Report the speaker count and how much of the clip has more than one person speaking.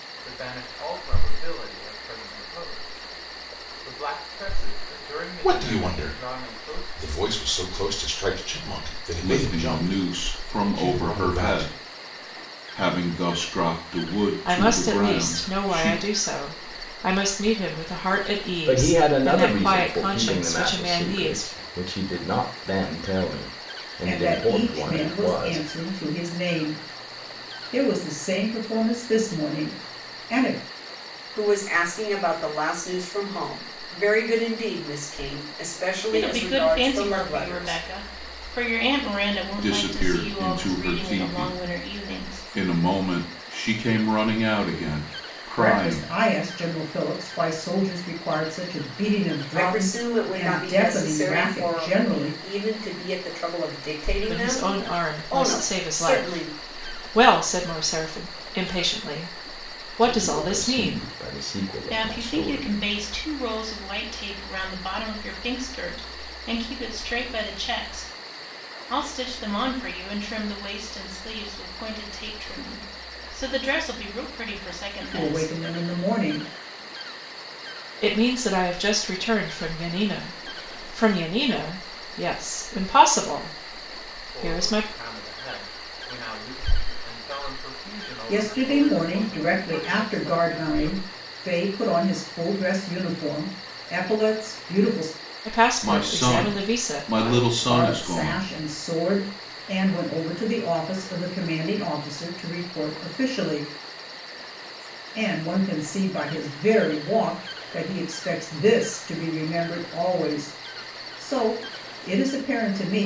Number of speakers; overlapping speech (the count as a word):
eight, about 26%